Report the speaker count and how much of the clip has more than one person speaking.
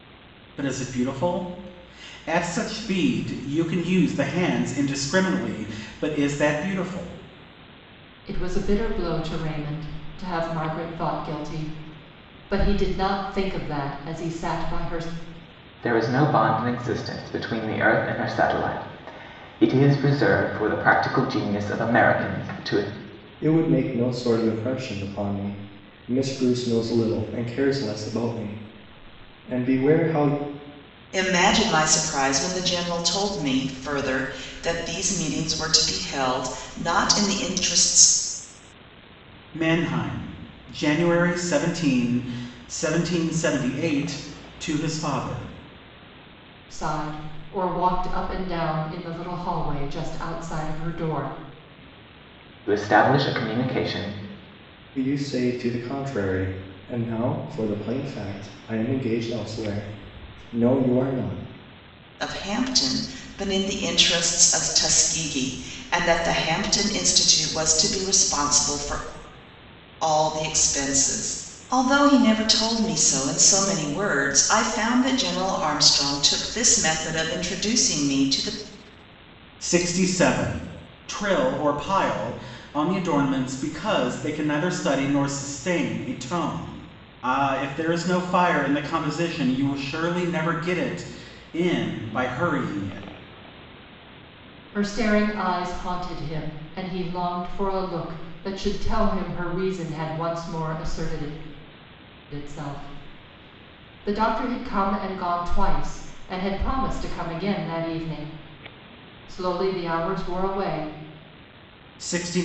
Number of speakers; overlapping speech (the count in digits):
5, no overlap